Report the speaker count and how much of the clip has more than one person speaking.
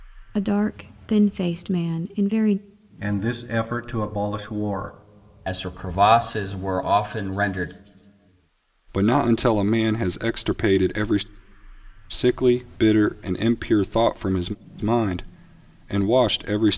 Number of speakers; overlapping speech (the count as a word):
four, no overlap